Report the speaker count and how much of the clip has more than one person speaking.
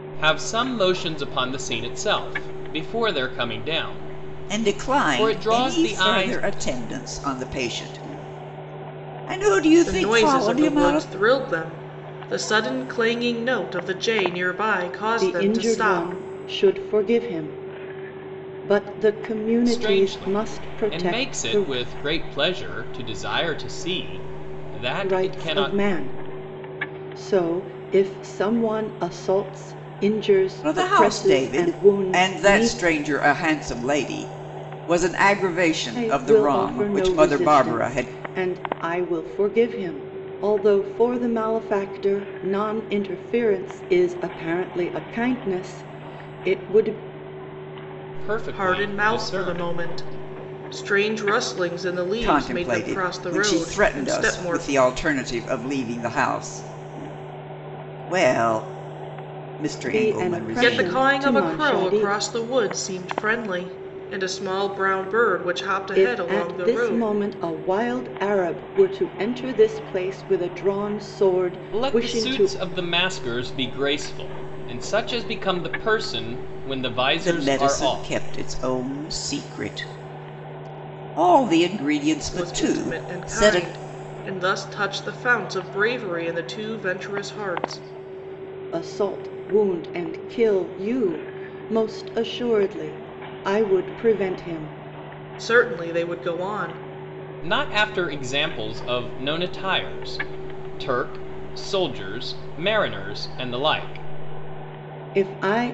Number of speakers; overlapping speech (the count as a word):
four, about 20%